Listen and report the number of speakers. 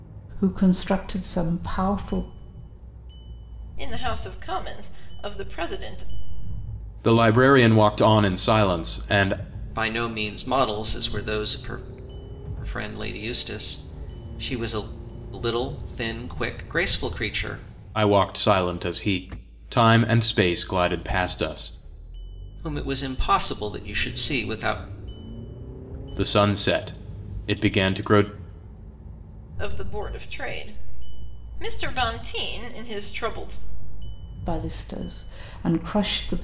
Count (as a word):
four